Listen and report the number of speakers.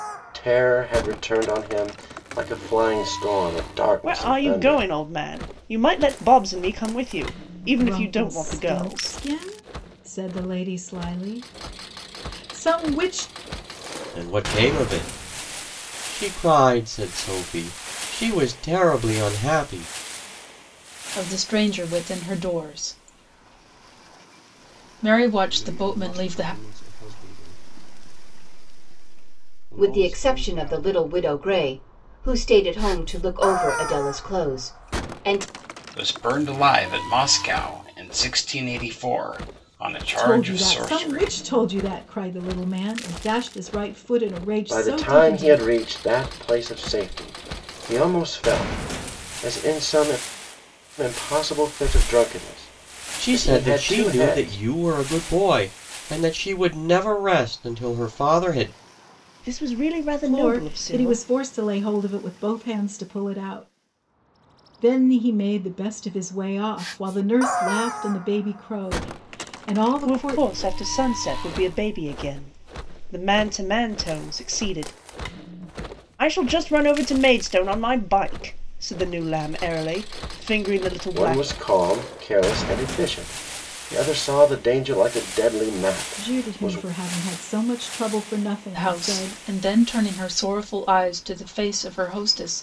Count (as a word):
eight